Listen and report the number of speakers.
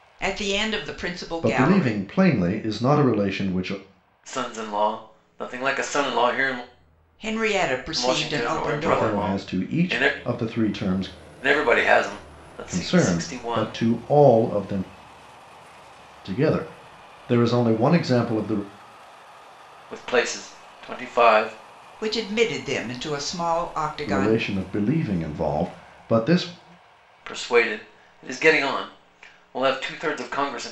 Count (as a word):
three